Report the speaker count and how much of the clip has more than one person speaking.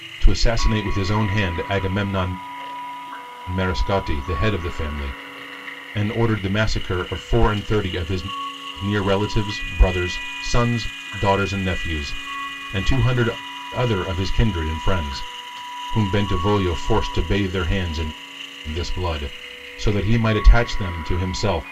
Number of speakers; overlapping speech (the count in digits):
1, no overlap